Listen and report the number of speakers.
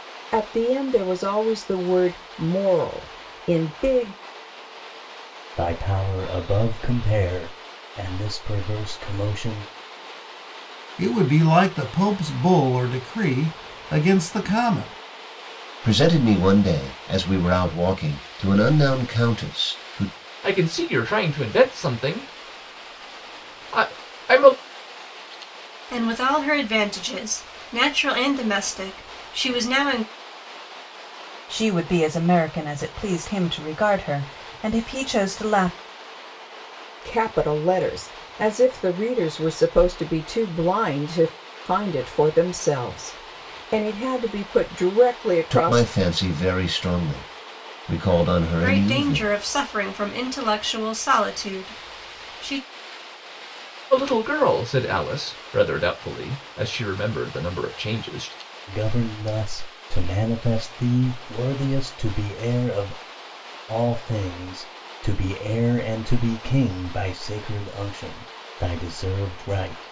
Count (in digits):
7